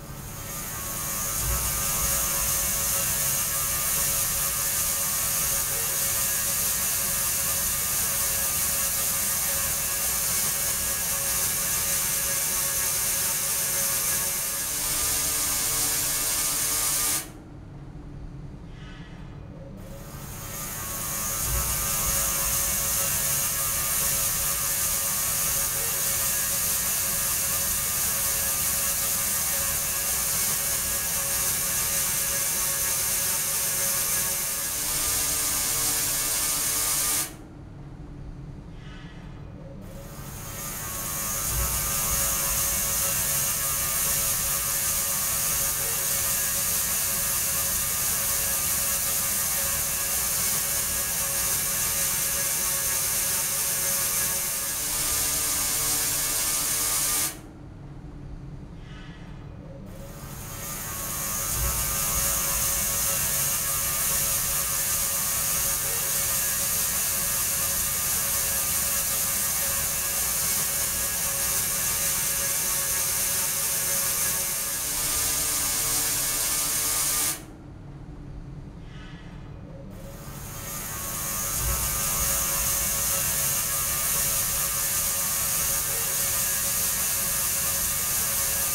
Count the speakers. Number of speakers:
zero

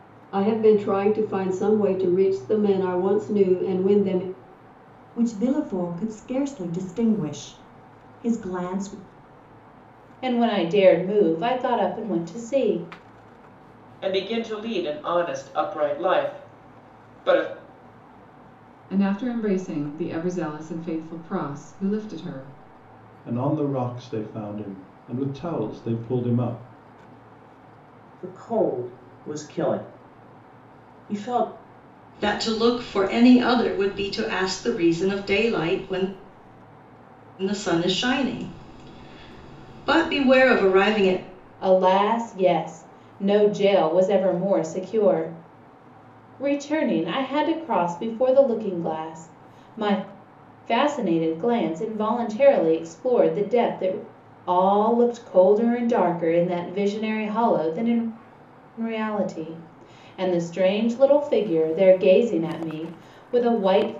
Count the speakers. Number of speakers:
eight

